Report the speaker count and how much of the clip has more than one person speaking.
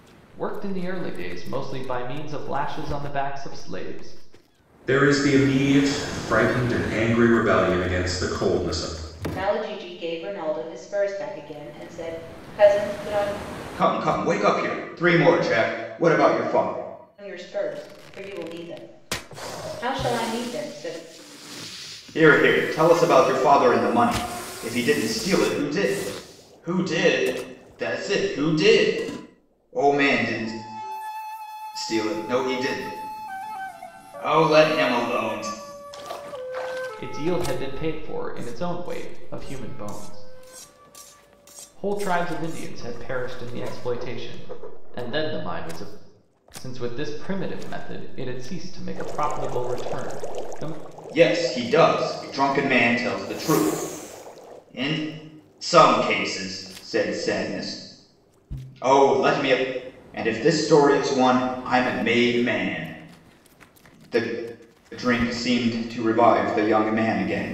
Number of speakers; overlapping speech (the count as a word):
four, no overlap